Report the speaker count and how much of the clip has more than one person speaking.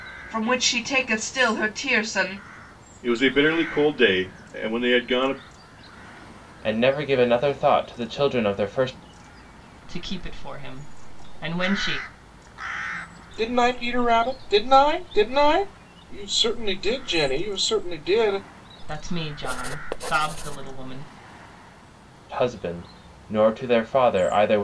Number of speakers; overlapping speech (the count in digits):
5, no overlap